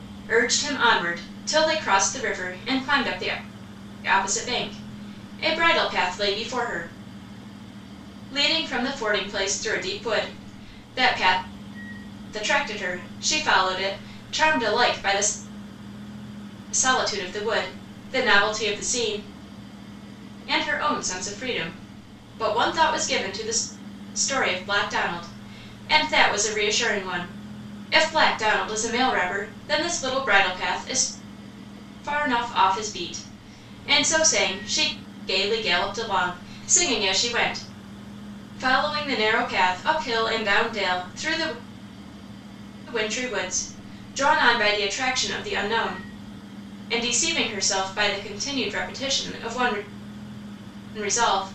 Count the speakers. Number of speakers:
one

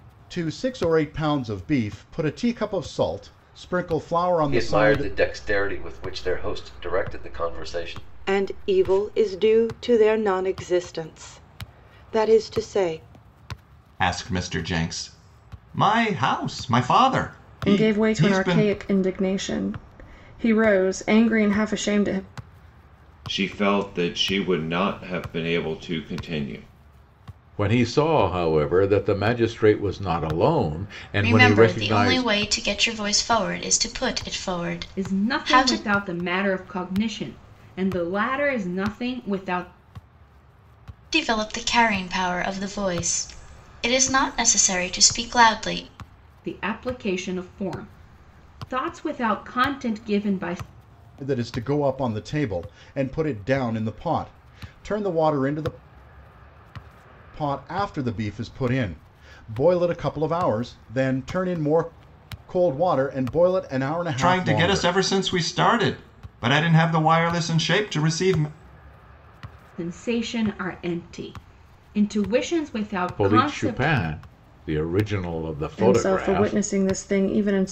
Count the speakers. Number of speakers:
nine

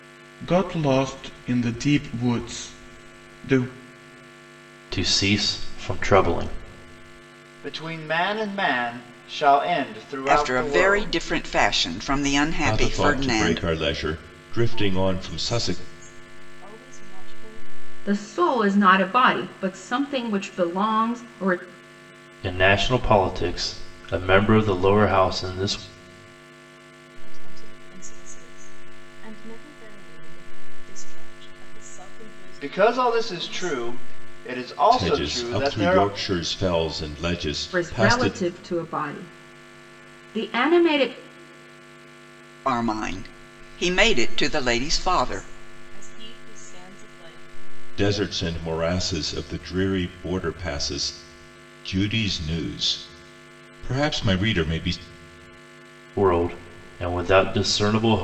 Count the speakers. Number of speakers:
seven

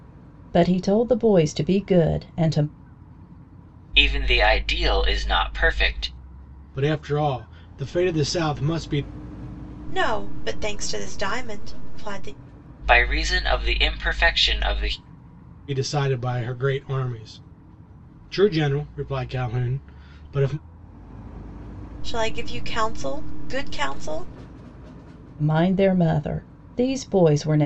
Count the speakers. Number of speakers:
four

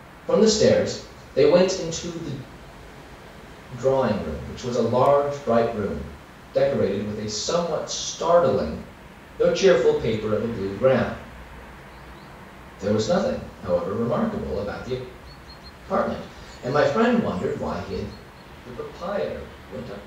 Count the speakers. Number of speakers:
one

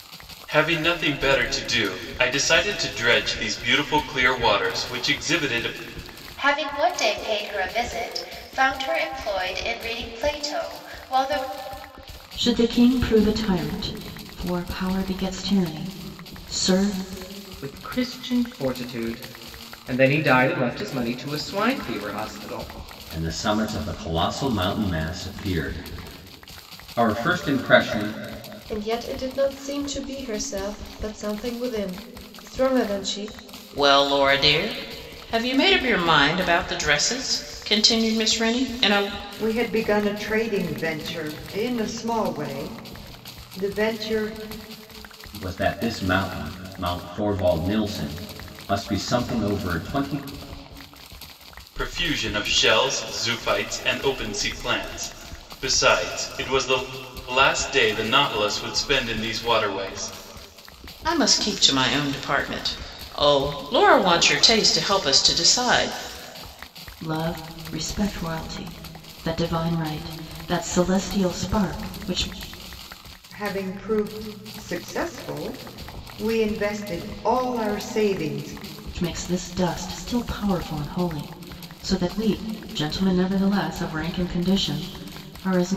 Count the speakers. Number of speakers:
eight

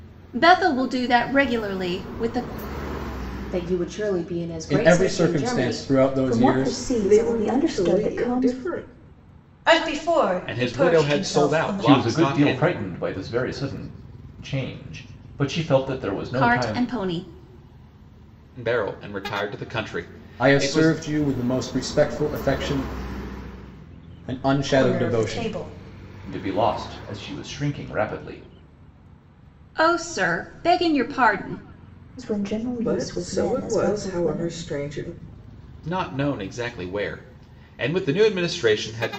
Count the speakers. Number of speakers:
eight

